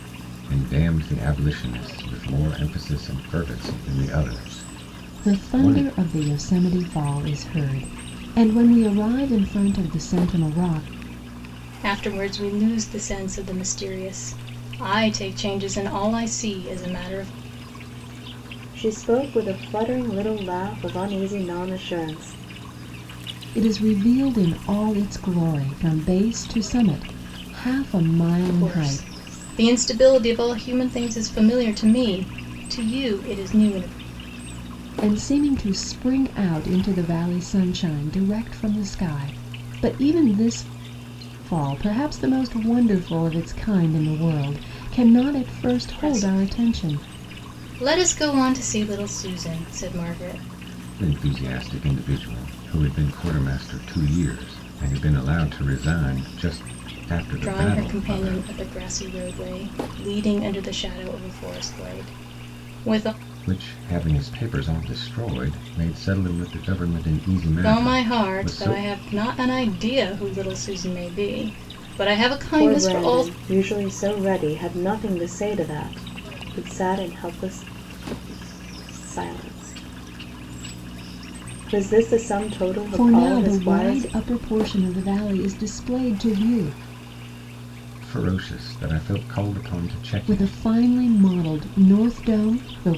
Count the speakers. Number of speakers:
4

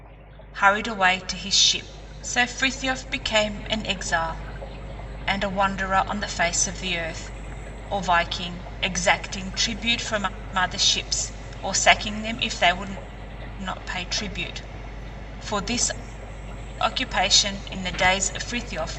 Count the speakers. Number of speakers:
1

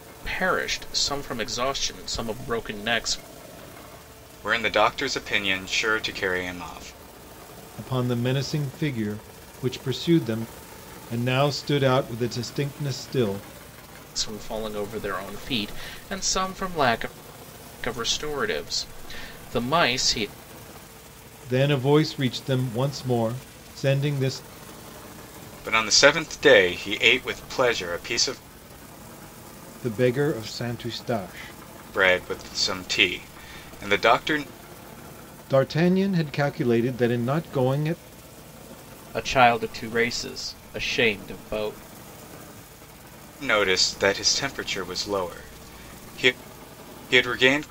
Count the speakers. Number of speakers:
3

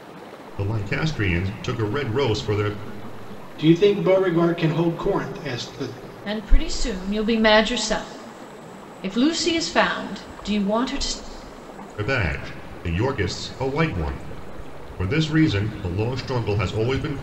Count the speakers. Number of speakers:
3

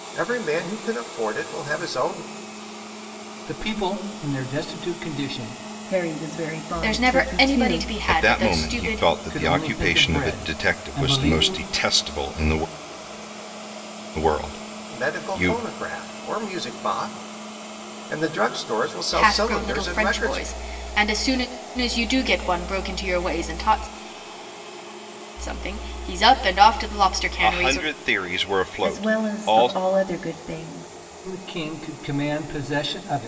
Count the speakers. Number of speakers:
5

